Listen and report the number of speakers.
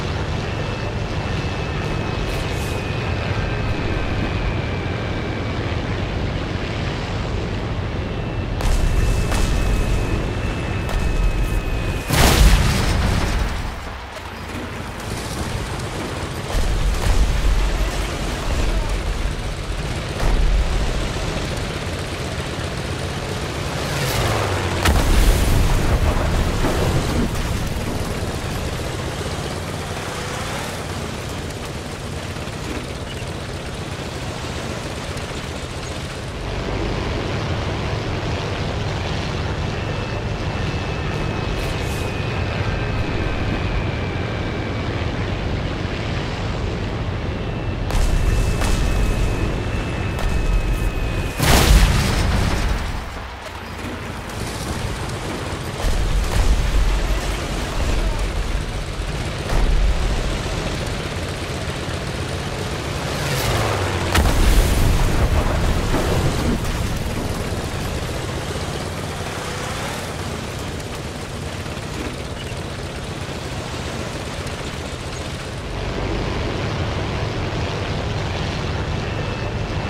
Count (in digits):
0